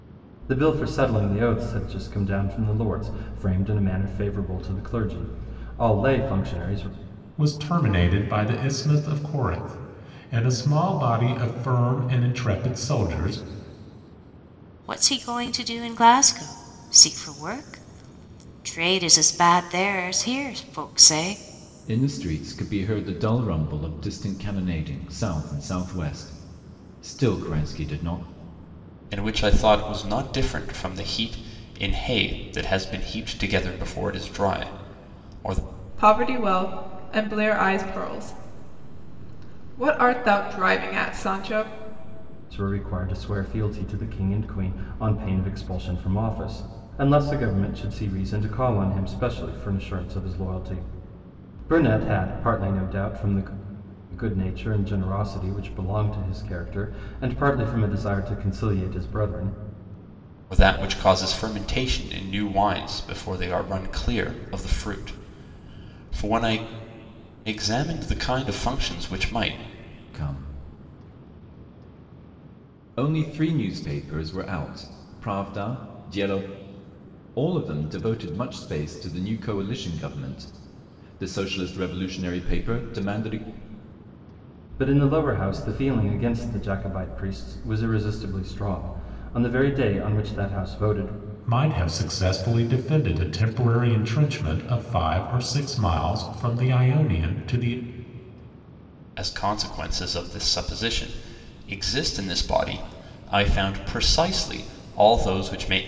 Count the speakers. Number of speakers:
6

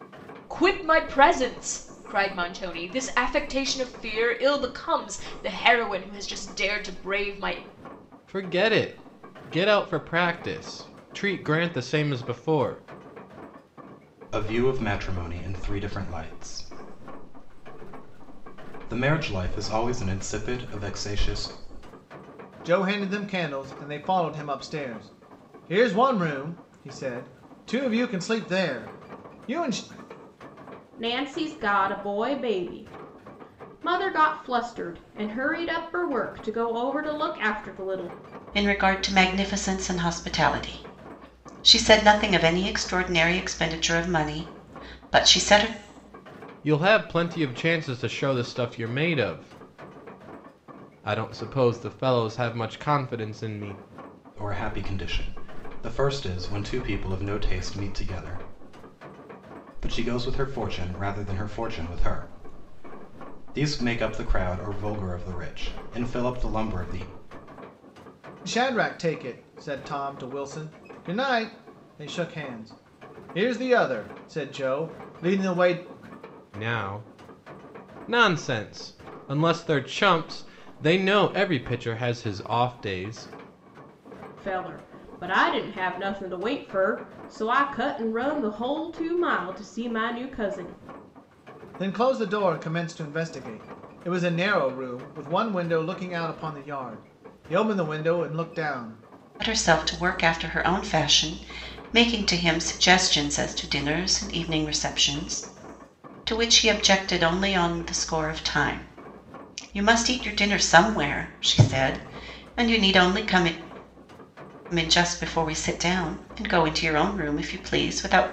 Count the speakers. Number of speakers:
6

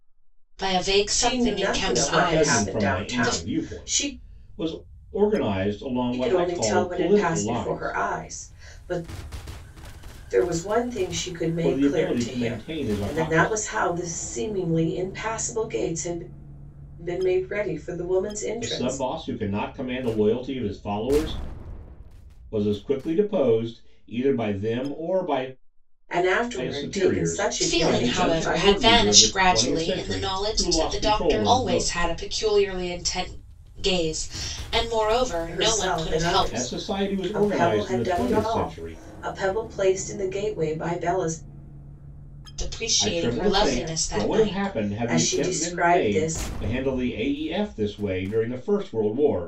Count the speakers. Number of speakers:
3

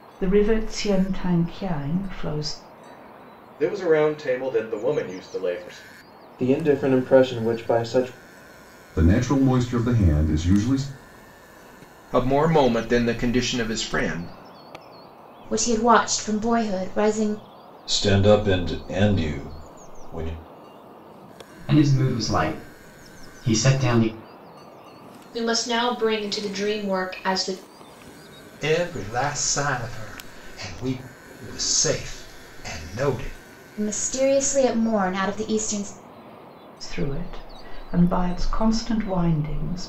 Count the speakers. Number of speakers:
10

